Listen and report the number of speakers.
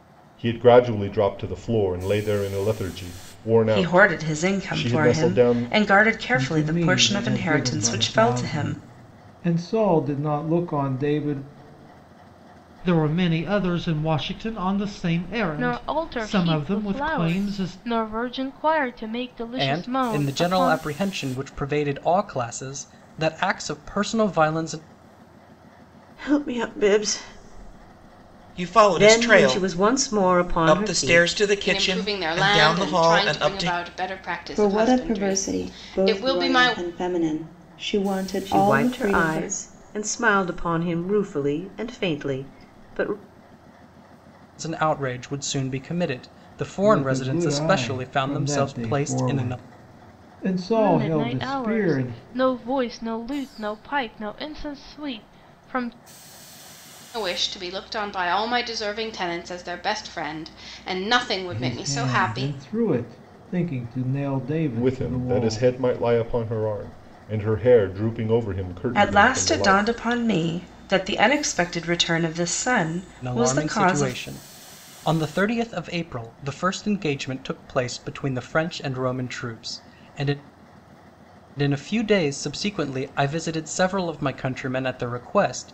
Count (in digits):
10